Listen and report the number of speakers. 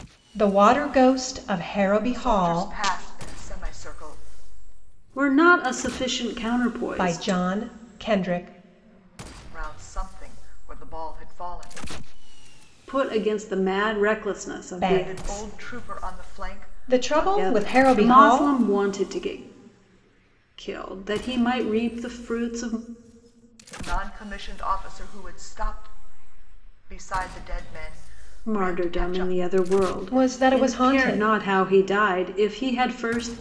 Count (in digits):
3